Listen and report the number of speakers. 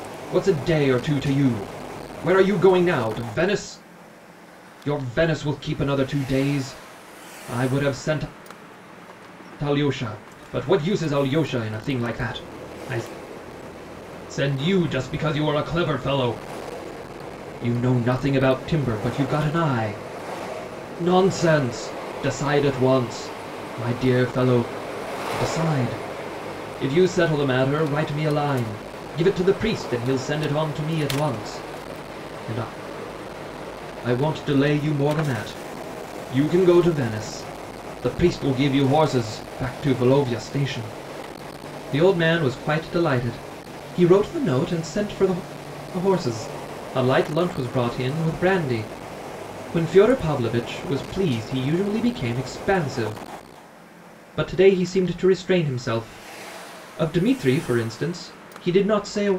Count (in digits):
1